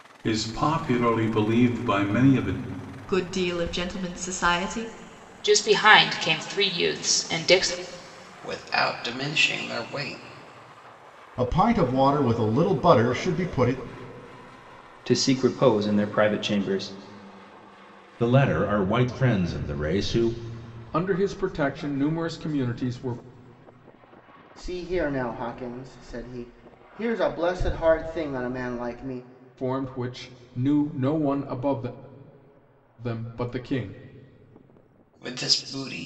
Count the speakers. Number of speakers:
nine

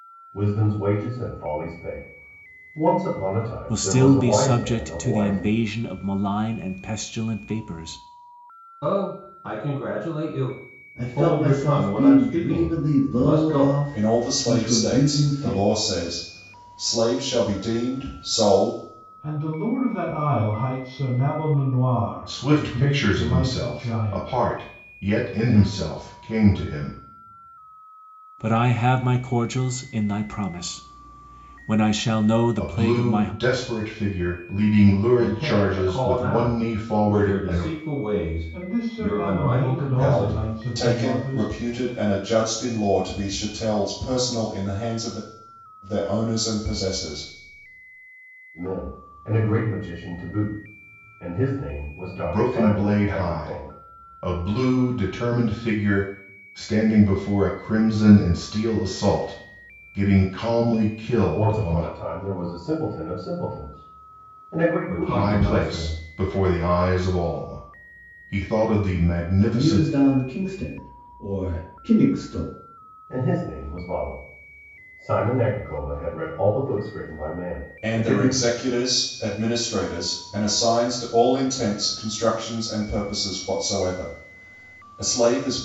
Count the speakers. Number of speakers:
seven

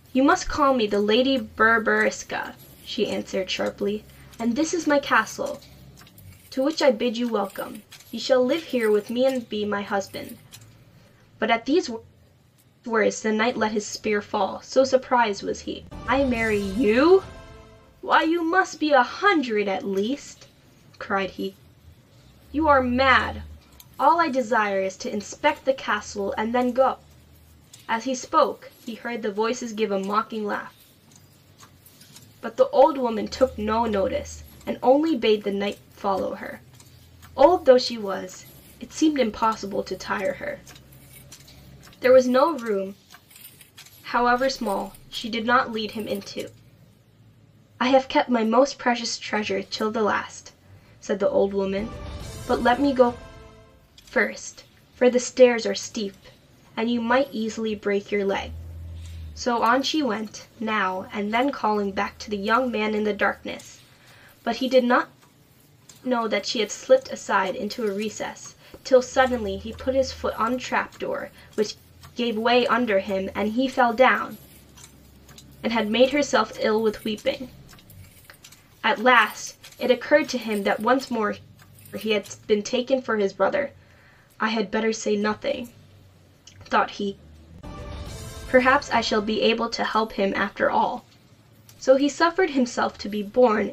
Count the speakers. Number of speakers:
one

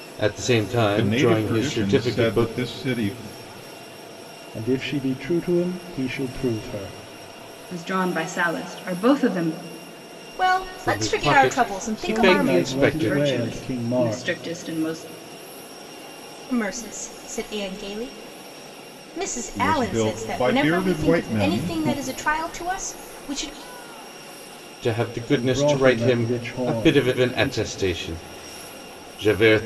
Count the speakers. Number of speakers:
five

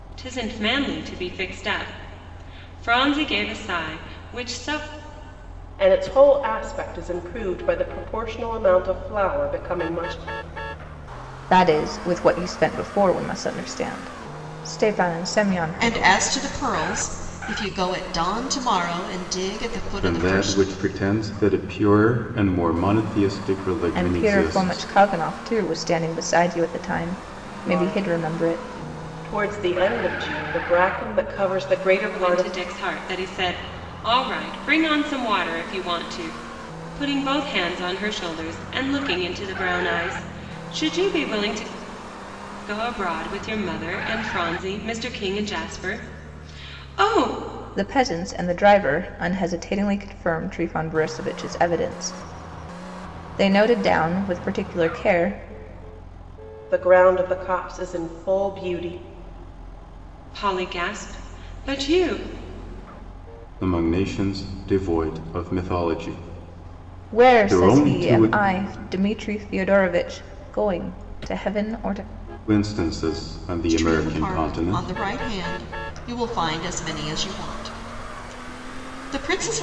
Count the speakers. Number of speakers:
five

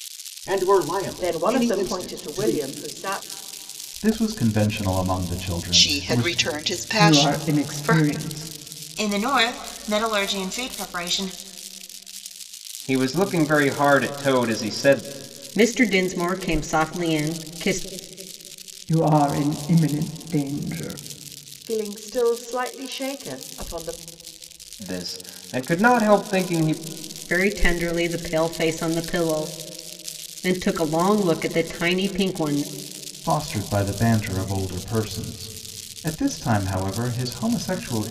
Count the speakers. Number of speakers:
eight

